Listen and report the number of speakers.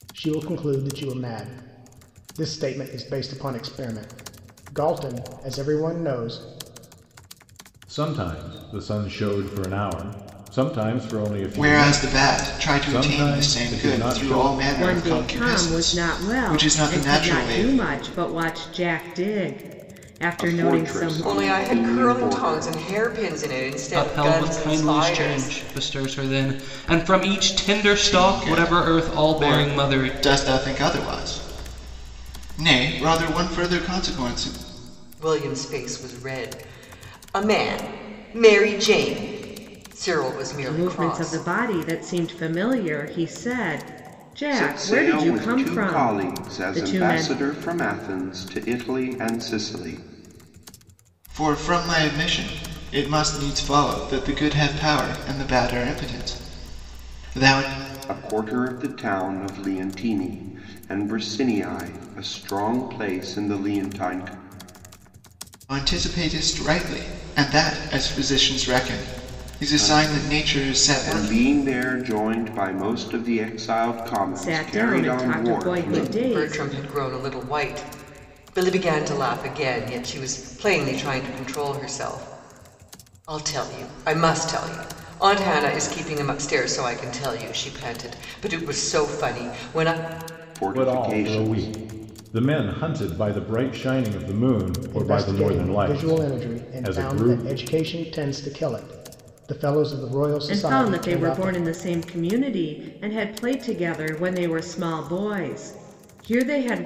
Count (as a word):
seven